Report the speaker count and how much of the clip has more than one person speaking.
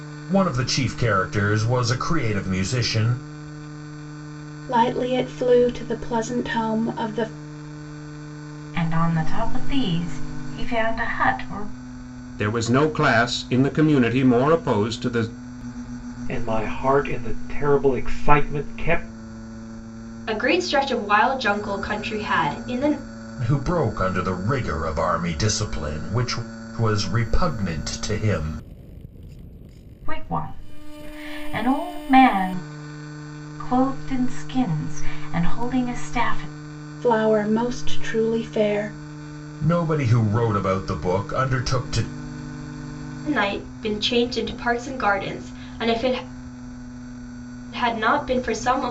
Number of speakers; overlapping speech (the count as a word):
six, no overlap